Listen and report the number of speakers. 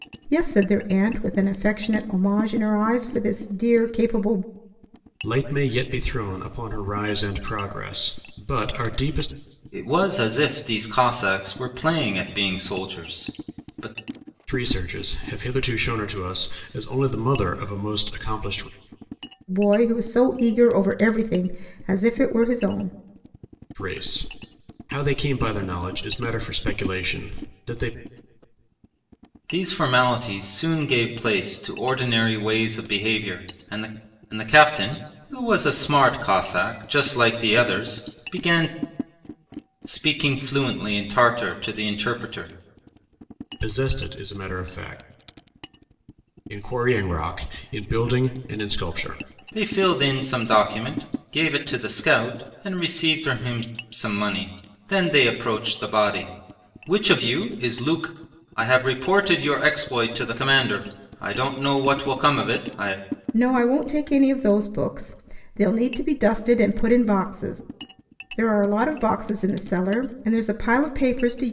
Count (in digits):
3